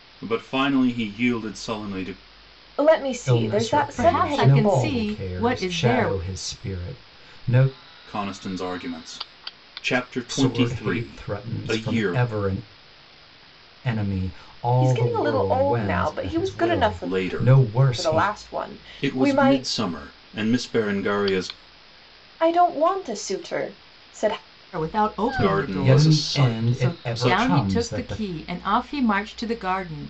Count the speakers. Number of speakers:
four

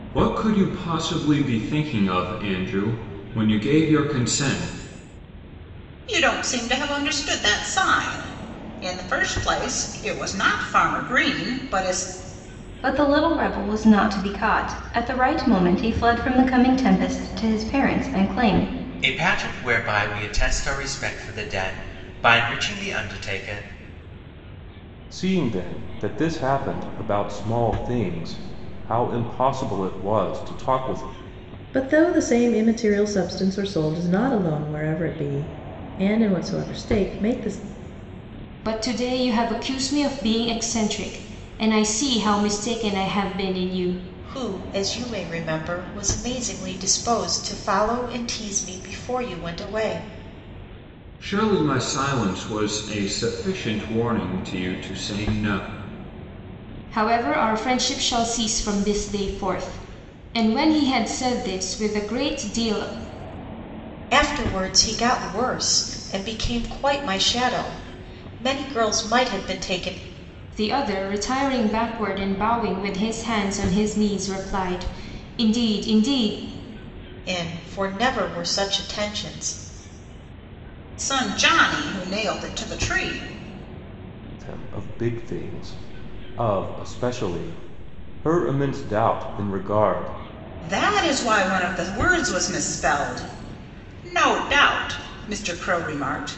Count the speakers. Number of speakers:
eight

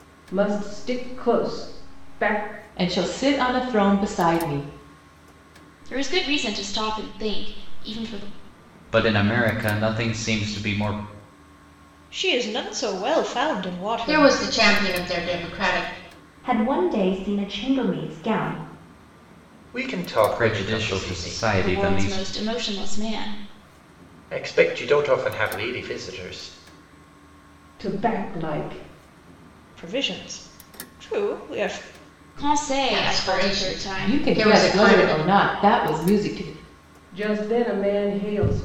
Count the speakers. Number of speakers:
eight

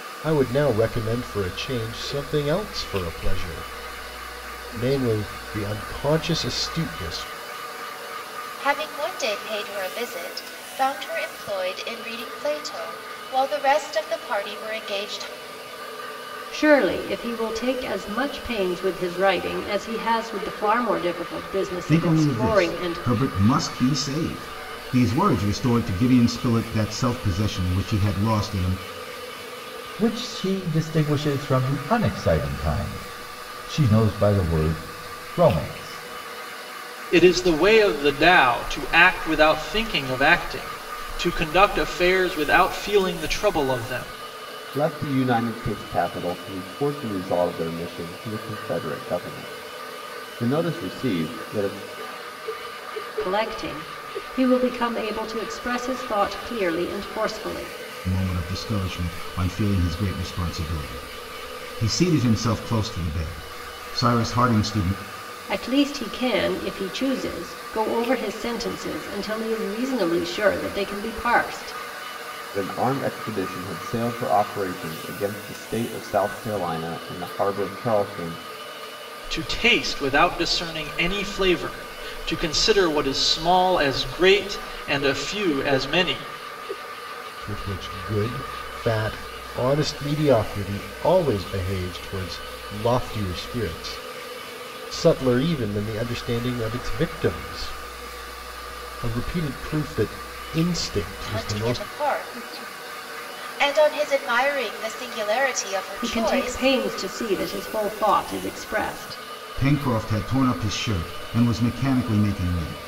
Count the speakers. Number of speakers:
seven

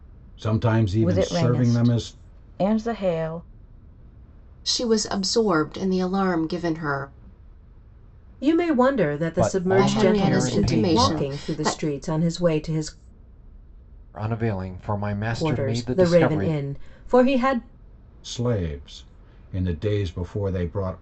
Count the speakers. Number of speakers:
five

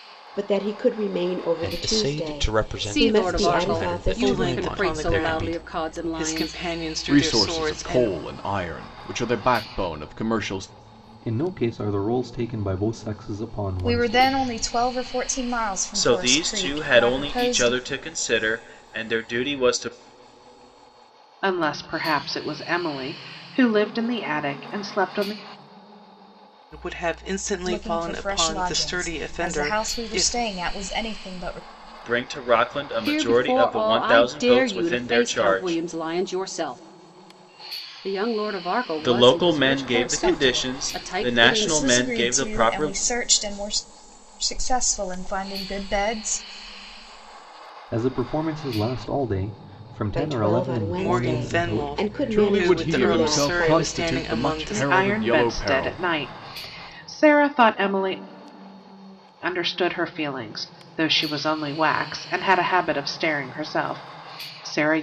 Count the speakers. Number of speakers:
nine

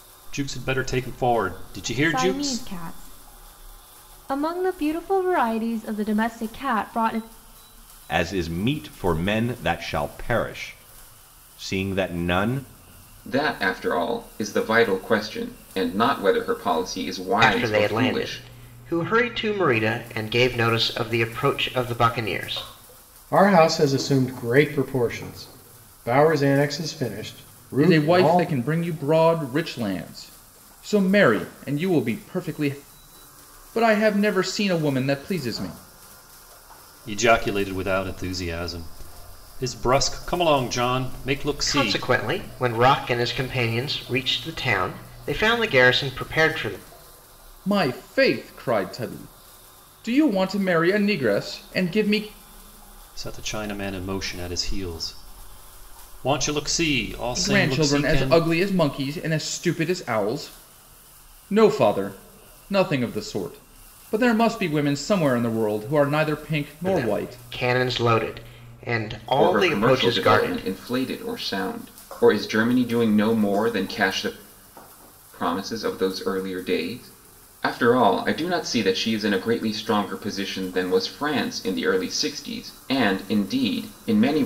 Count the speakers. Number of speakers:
seven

